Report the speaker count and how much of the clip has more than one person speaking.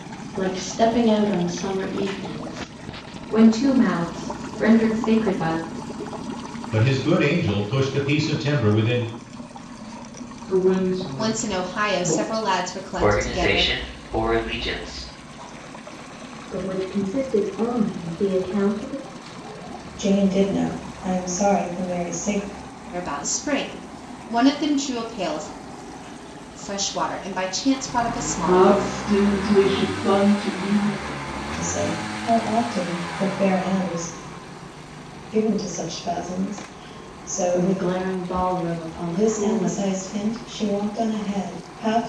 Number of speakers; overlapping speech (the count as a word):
eight, about 8%